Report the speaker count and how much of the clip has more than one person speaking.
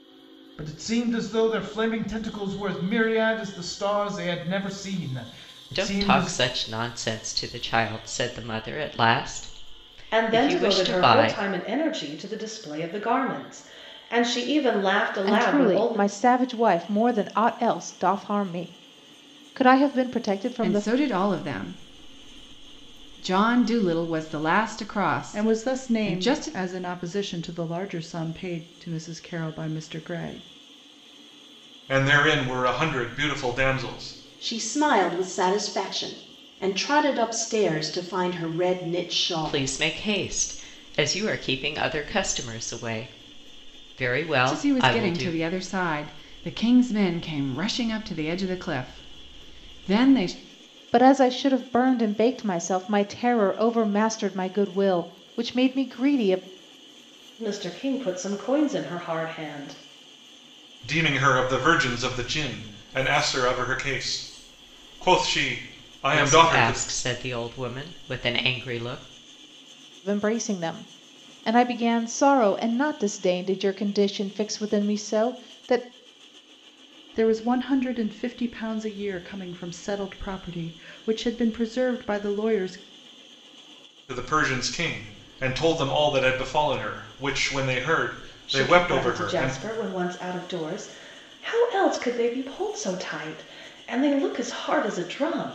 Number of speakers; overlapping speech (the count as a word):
eight, about 8%